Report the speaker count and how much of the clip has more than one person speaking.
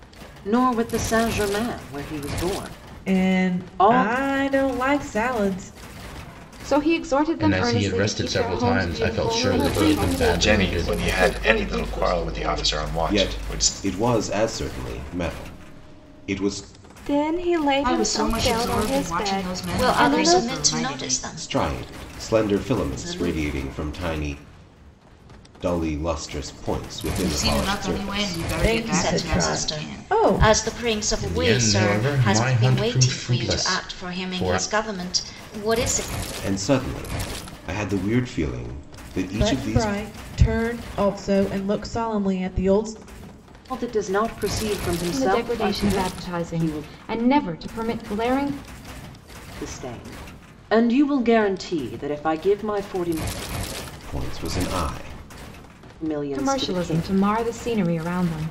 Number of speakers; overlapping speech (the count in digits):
10, about 38%